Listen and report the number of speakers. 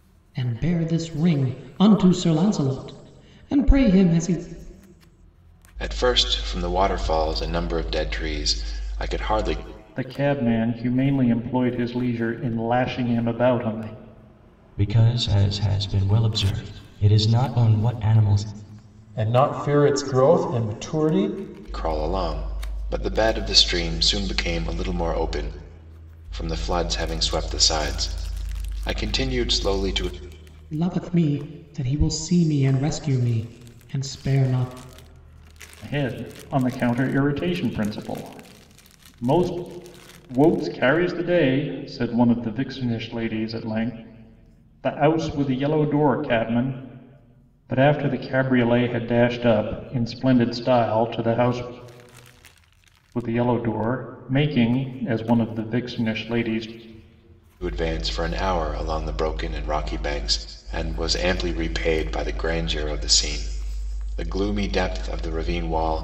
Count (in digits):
5